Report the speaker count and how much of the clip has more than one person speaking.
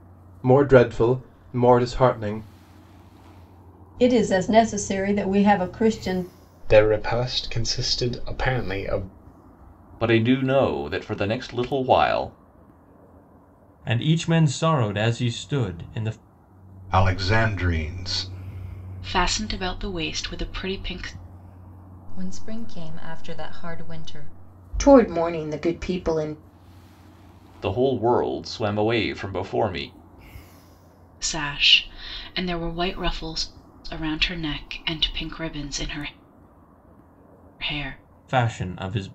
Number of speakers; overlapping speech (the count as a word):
nine, no overlap